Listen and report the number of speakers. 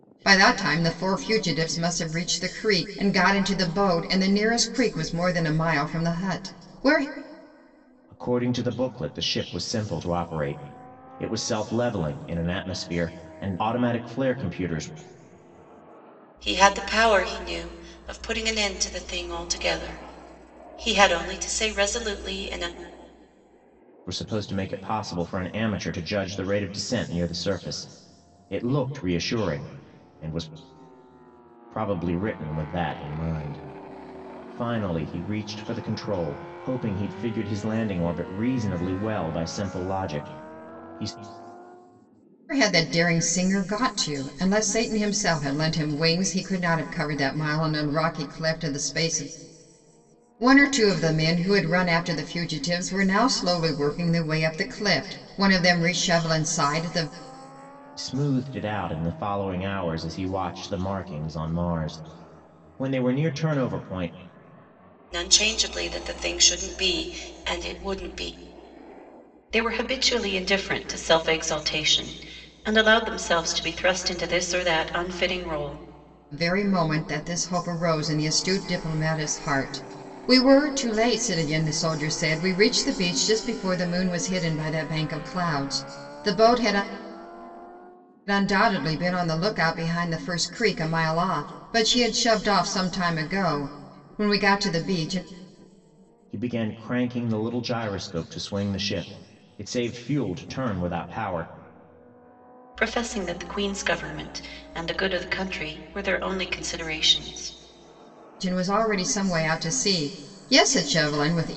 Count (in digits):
3